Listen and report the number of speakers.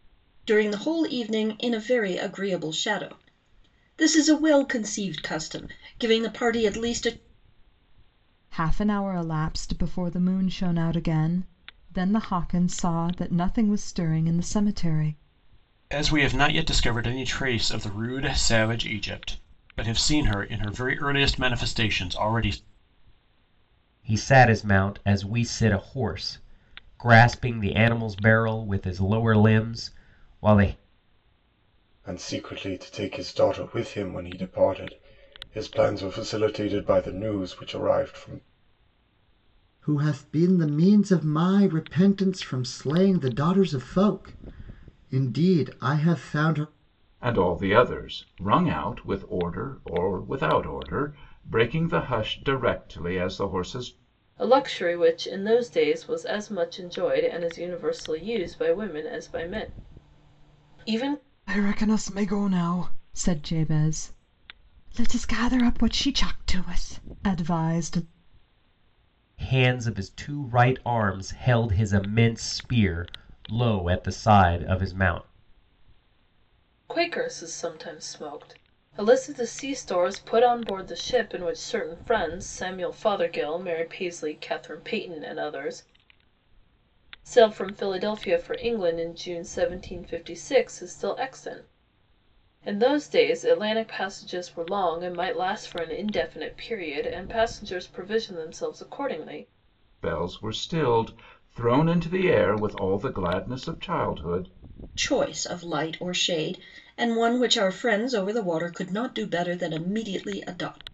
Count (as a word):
eight